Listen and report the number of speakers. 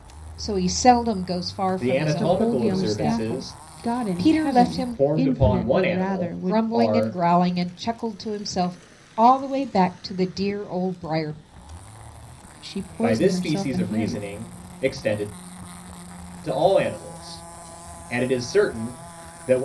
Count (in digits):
3